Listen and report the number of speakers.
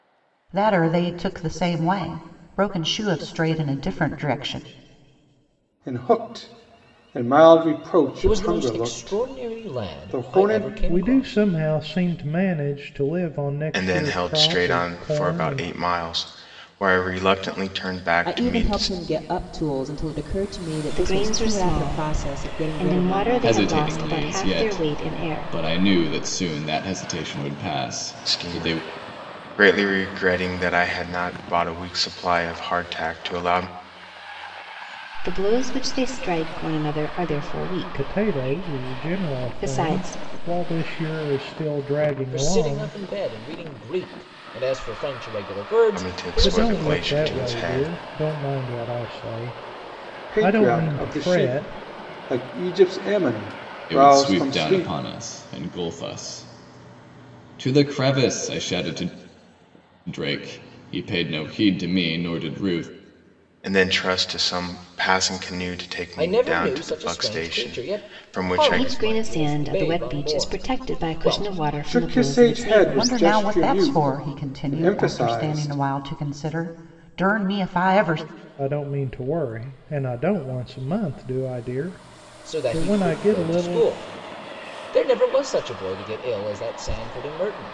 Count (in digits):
8